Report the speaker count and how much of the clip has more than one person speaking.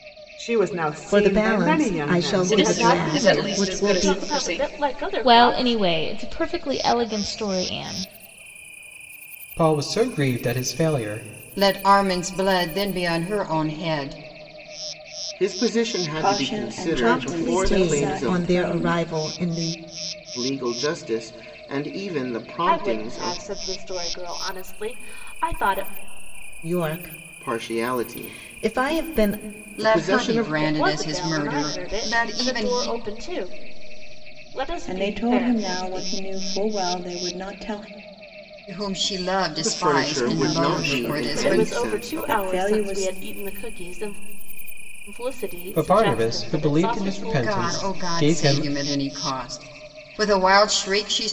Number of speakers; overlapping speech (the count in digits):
9, about 41%